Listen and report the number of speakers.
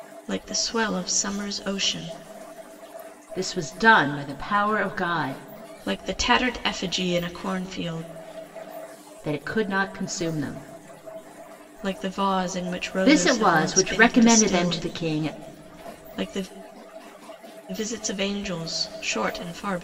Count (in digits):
2